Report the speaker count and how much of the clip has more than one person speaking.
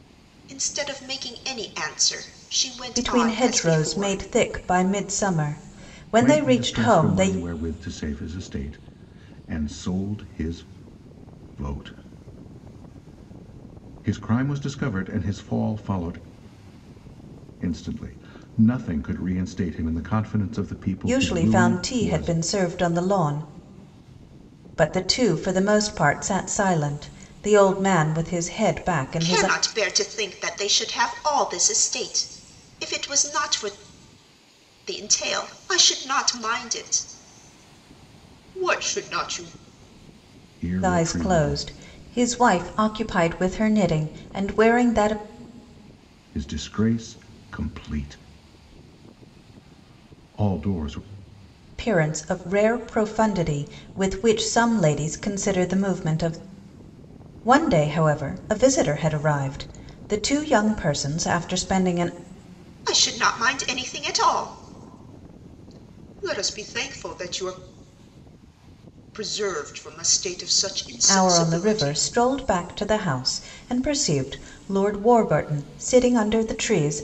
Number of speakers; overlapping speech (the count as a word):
three, about 8%